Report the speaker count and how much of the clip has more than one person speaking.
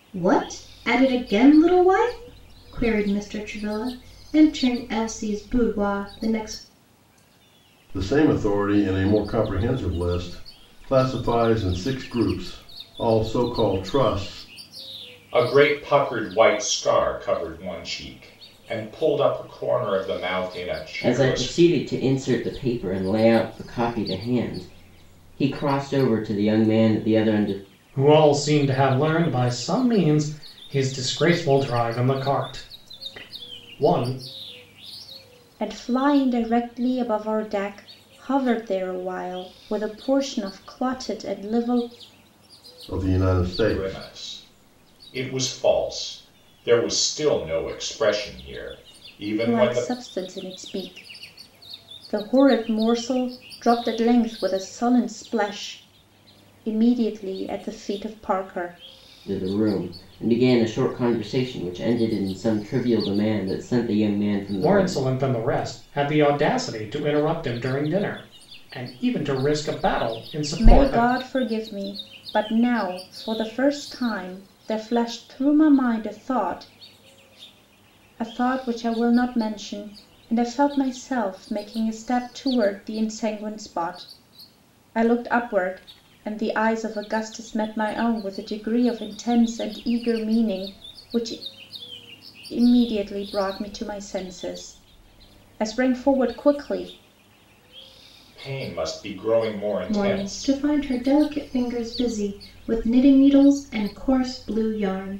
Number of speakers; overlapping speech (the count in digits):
6, about 3%